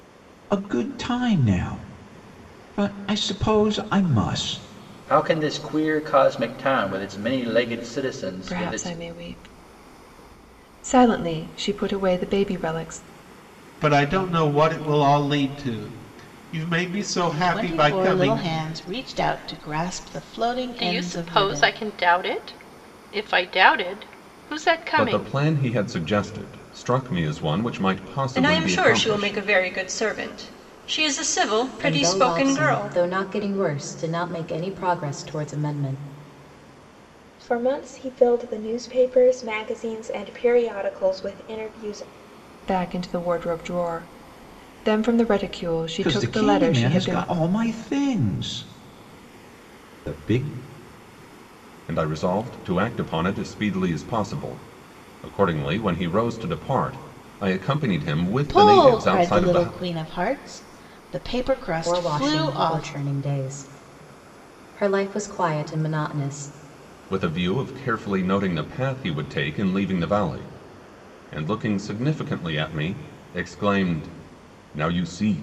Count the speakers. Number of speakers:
10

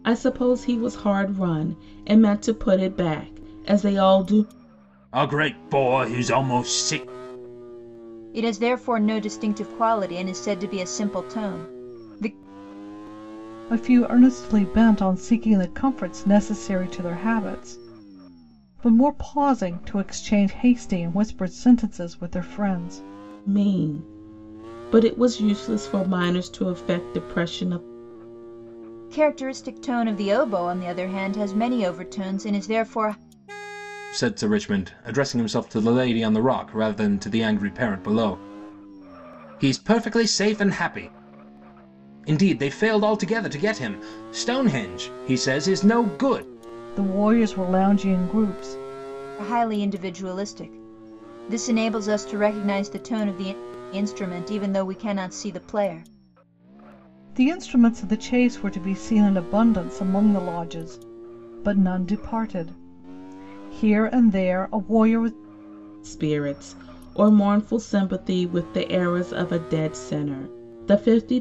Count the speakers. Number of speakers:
4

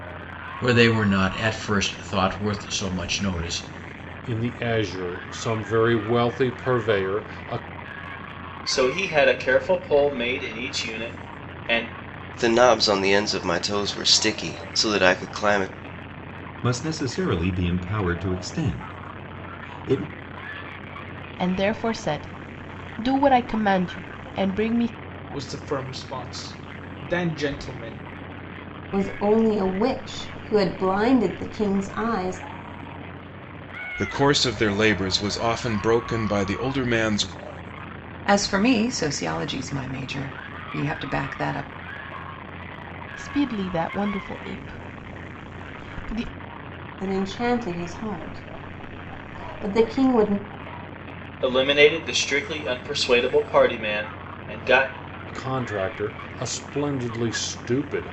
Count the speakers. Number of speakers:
10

